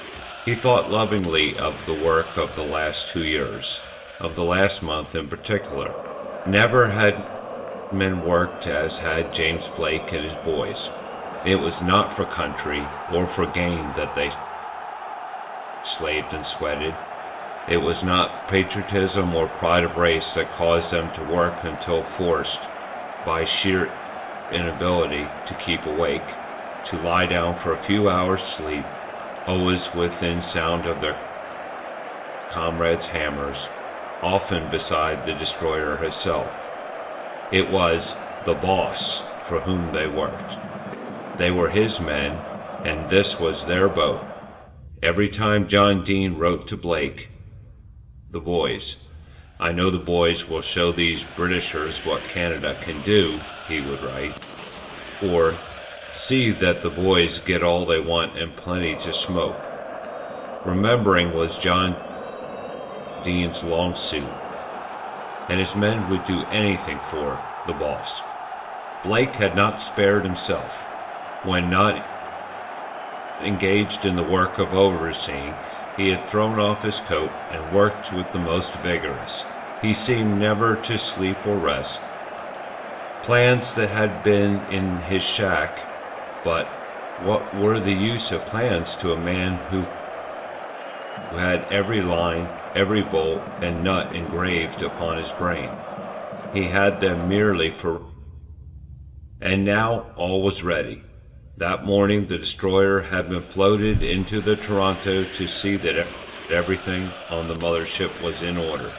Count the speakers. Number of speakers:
1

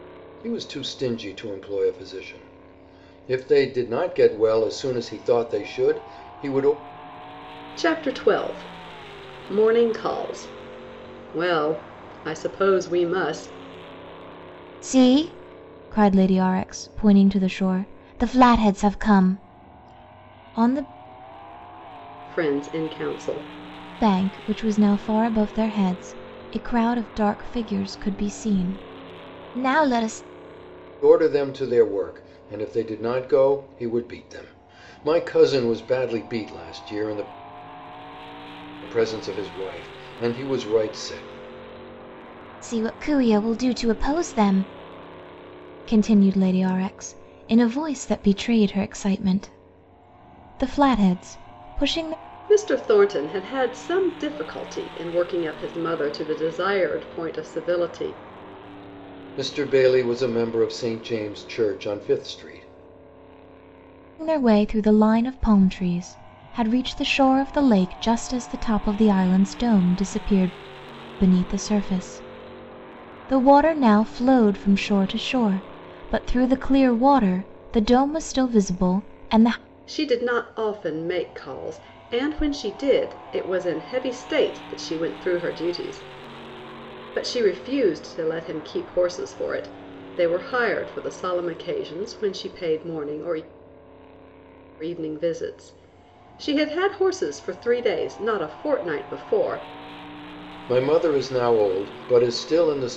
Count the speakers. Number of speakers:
3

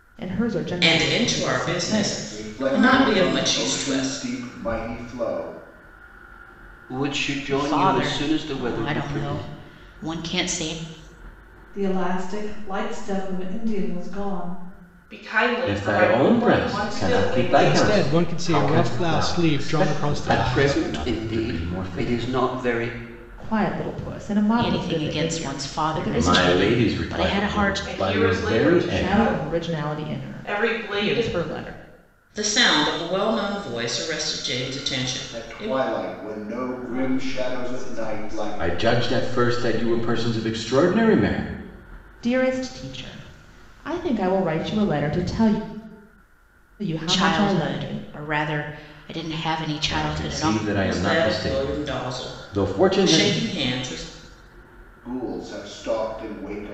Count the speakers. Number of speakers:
10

